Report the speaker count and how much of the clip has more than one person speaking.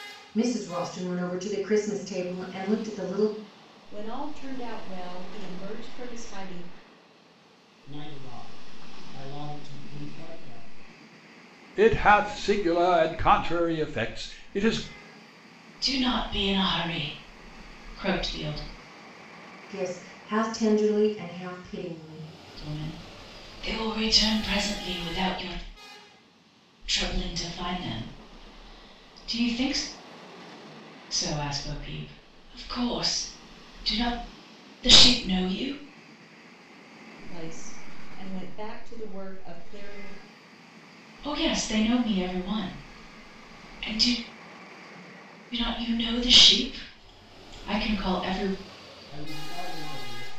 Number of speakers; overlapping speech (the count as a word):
five, no overlap